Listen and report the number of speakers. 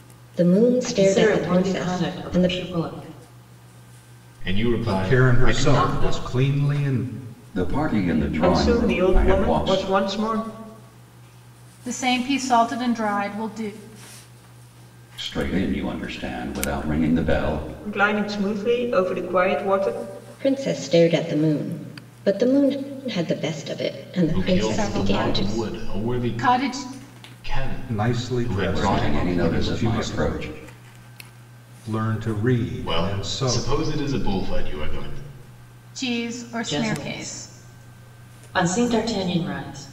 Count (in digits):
7